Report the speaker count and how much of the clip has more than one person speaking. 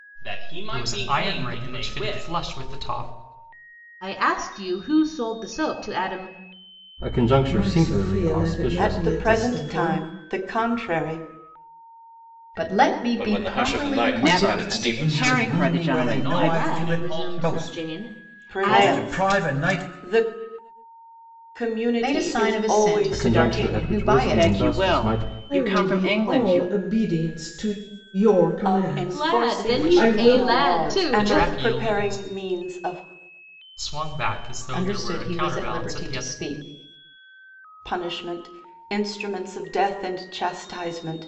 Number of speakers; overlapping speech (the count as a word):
ten, about 51%